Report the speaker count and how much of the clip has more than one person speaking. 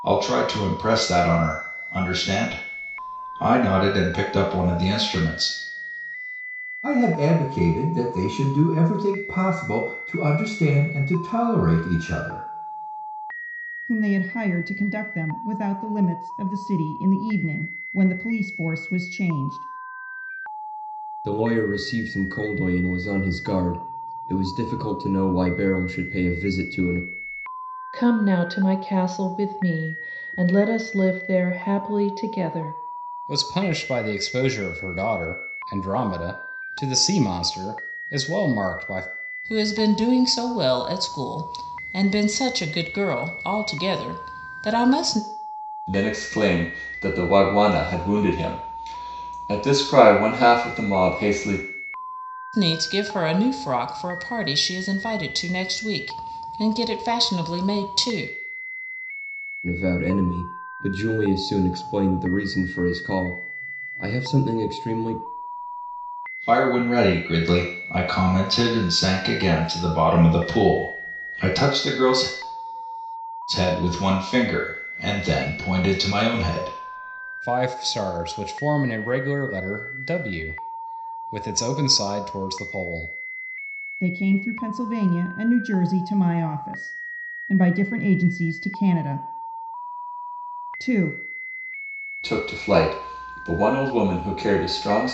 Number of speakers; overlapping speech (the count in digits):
8, no overlap